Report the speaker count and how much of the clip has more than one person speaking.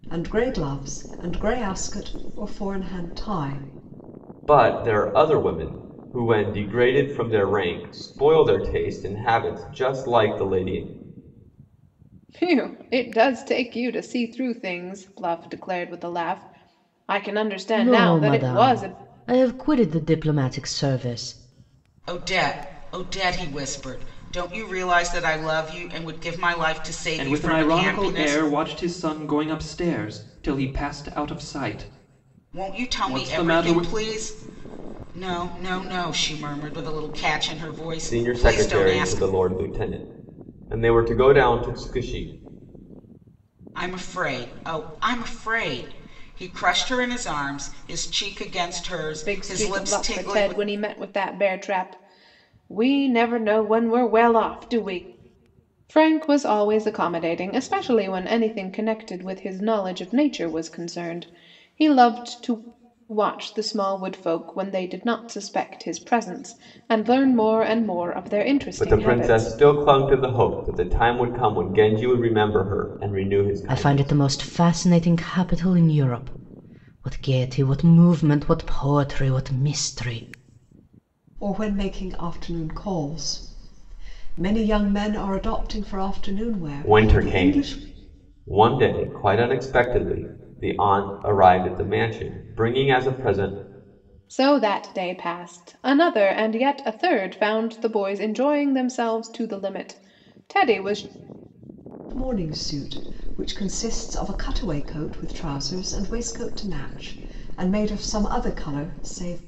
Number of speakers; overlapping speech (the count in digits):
6, about 8%